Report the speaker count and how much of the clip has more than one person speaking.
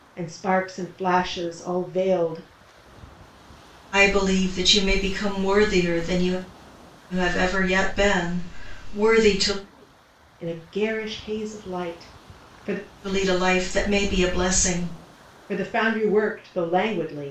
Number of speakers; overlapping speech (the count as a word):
two, no overlap